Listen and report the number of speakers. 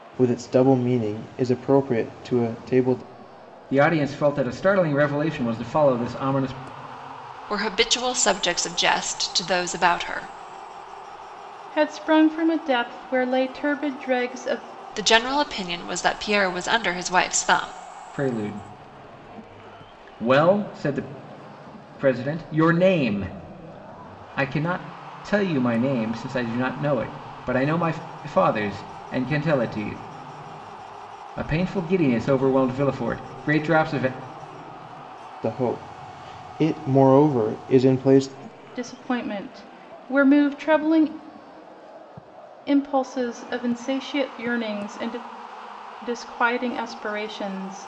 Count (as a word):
four